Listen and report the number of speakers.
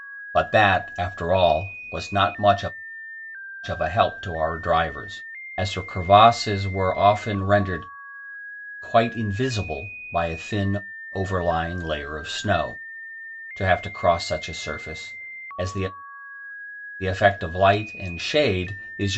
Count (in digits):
1